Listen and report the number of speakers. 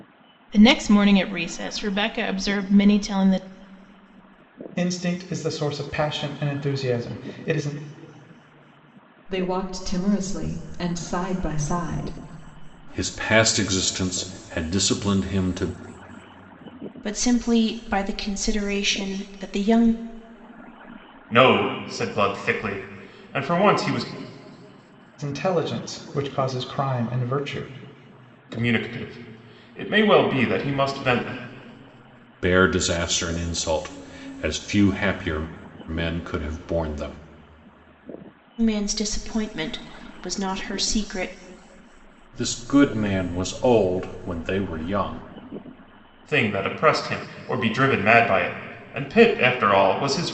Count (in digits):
6